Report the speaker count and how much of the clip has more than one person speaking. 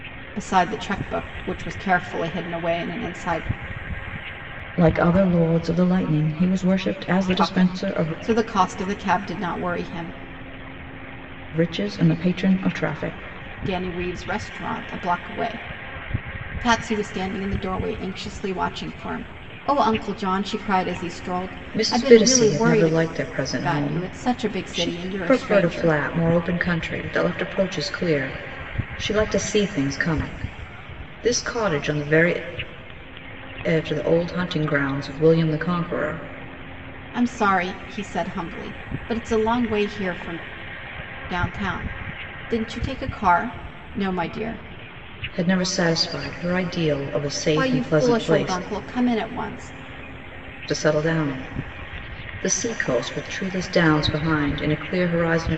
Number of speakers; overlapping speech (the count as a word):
two, about 10%